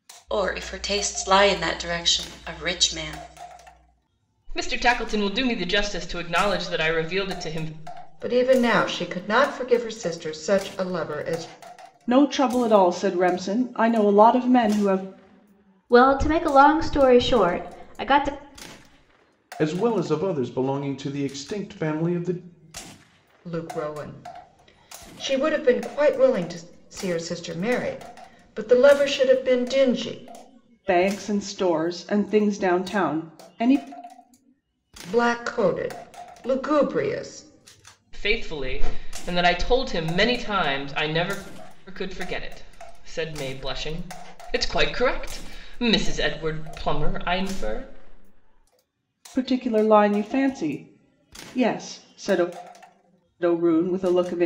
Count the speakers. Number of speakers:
six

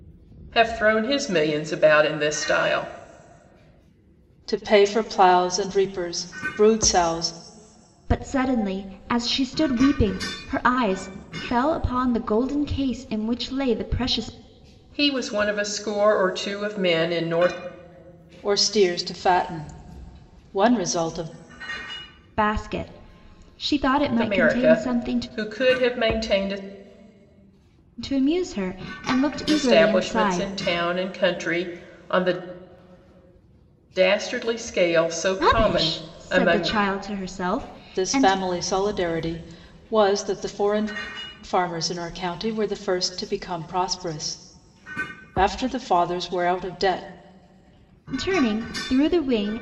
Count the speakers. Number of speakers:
three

